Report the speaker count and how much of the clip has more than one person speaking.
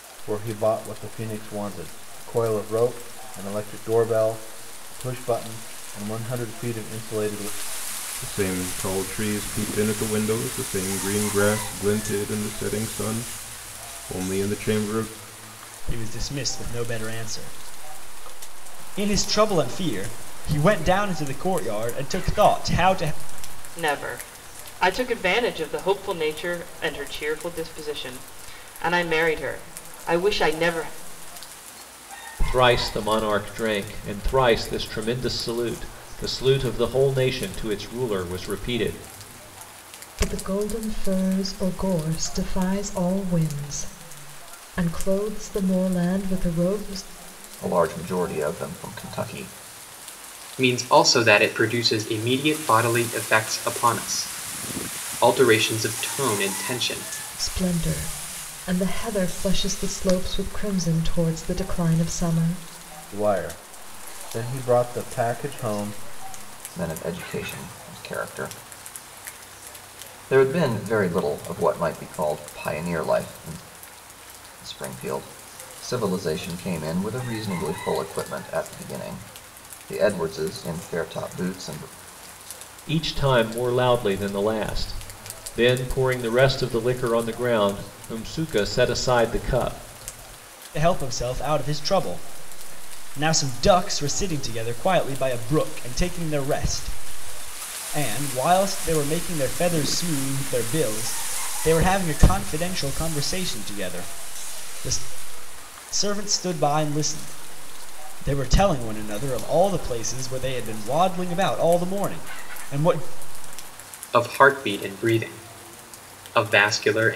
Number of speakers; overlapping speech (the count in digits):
8, no overlap